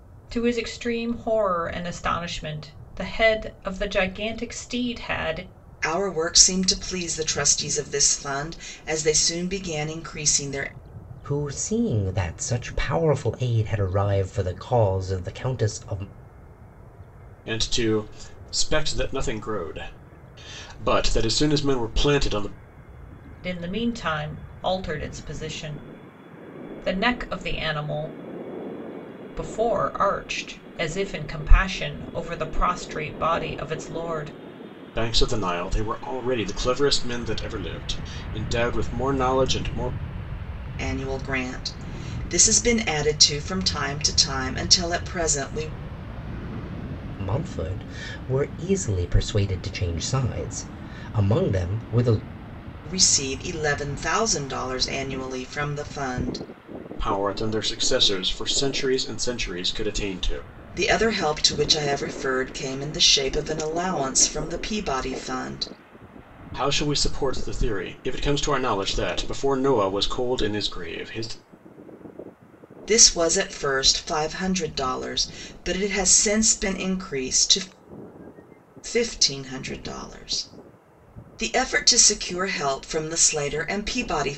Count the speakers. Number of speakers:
four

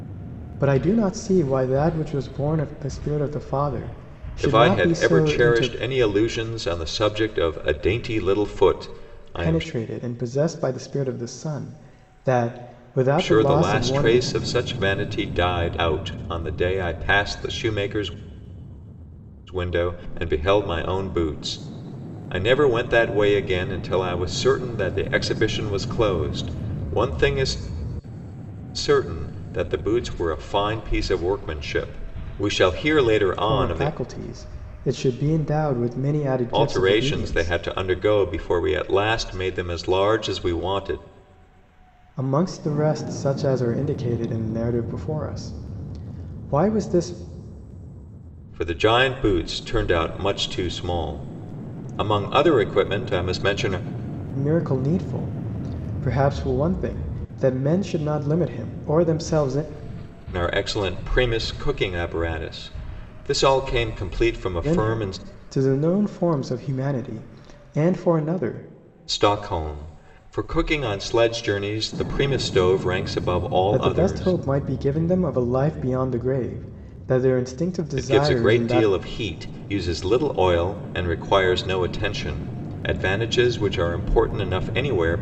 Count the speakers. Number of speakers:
two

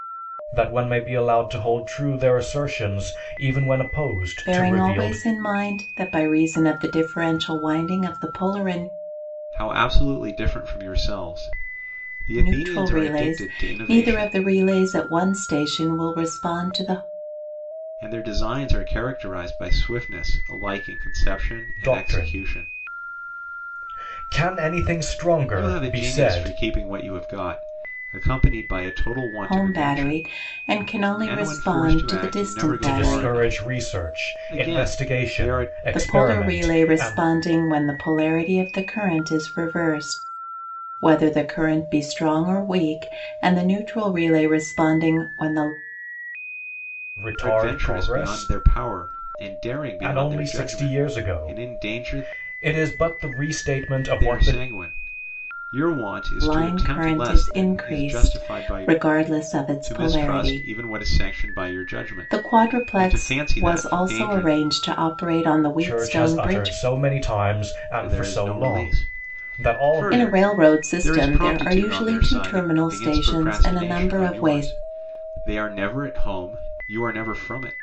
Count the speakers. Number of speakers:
three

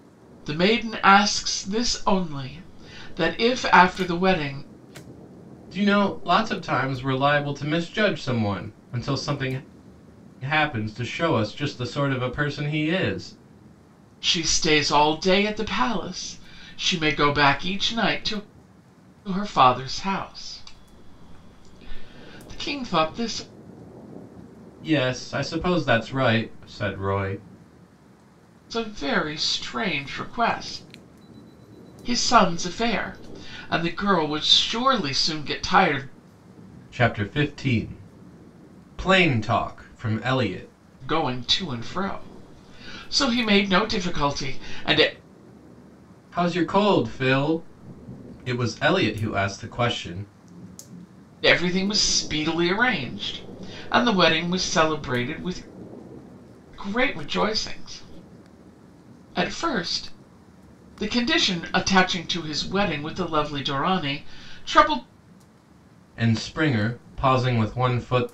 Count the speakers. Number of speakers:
two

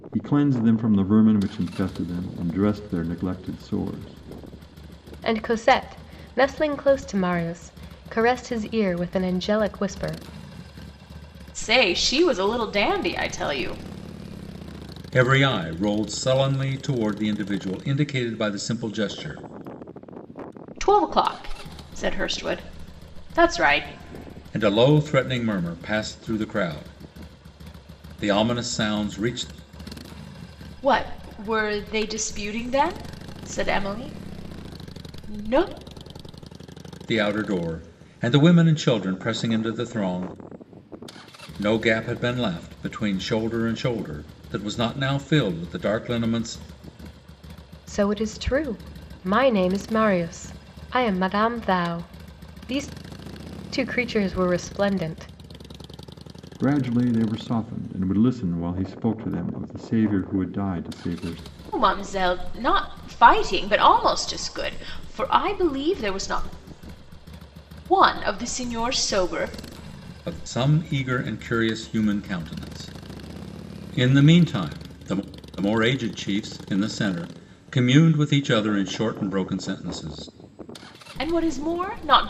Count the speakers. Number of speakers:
four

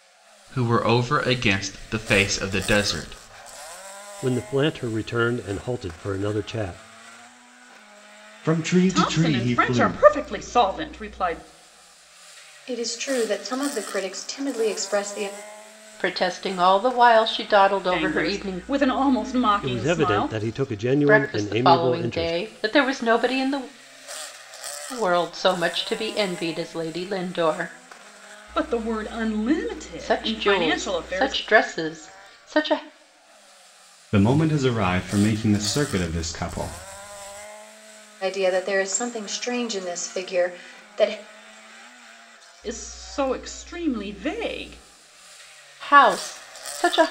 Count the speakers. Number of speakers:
six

